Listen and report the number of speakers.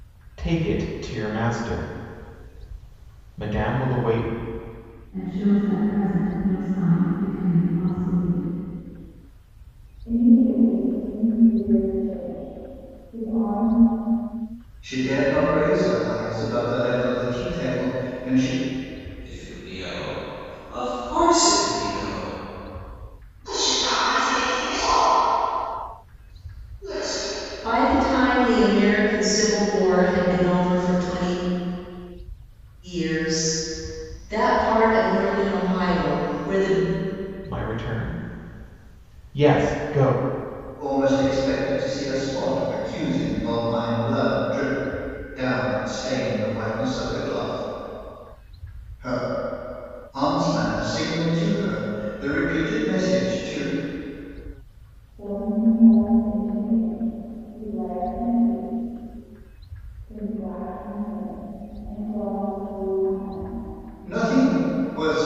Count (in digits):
7